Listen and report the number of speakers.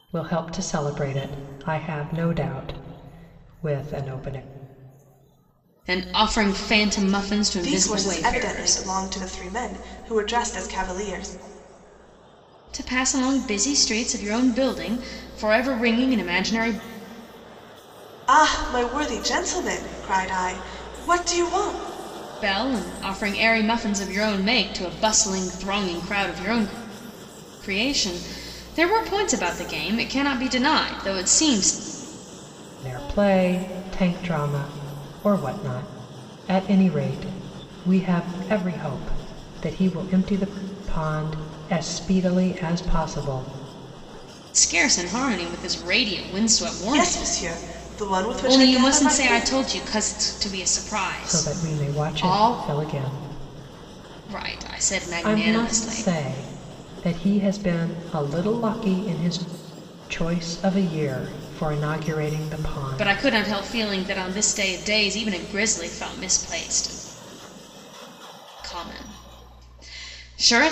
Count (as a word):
three